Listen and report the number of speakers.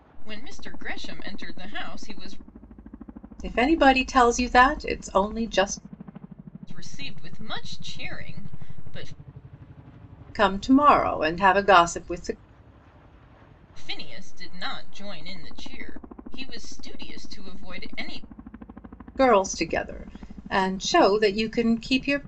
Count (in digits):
2